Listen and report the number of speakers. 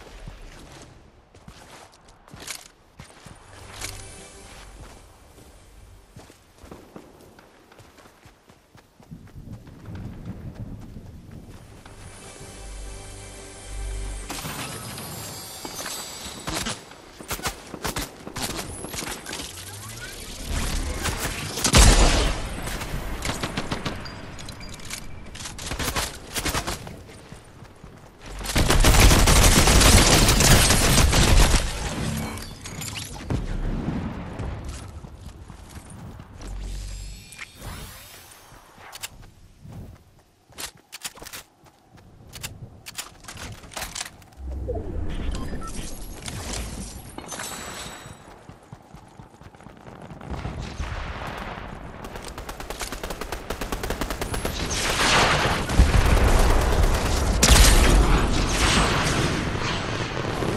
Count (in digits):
0